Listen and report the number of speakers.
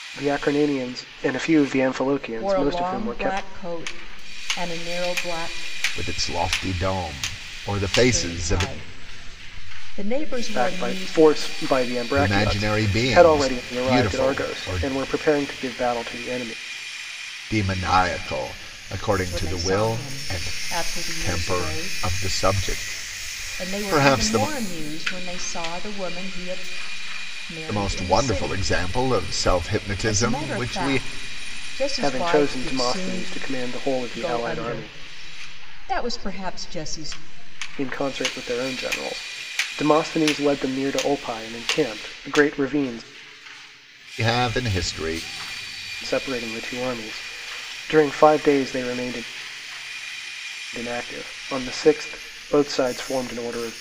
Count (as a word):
three